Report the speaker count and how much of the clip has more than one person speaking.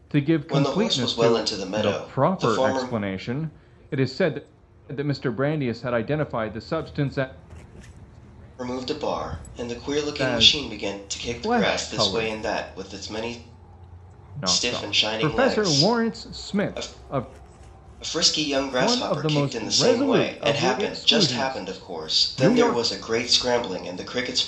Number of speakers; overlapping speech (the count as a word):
two, about 45%